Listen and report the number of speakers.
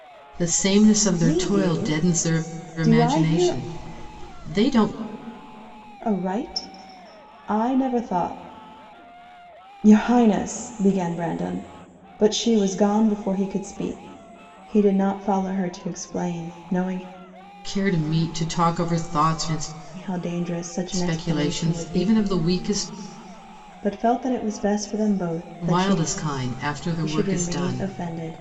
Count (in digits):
2